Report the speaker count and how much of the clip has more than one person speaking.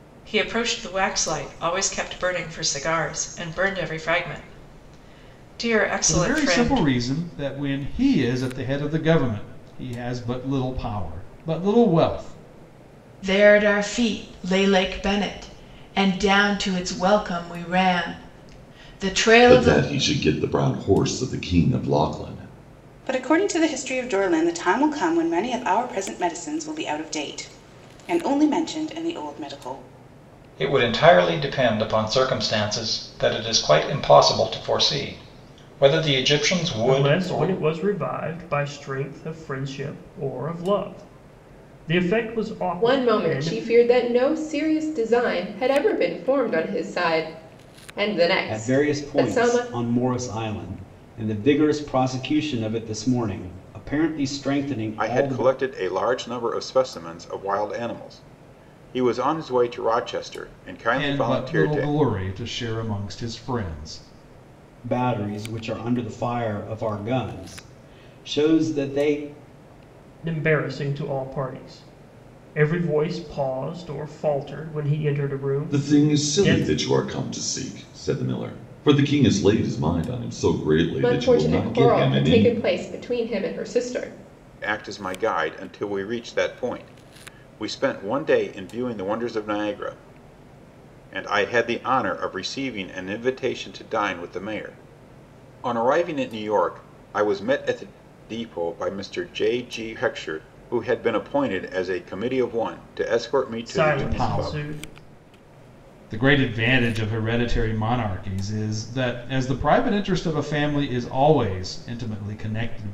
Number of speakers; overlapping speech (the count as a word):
ten, about 8%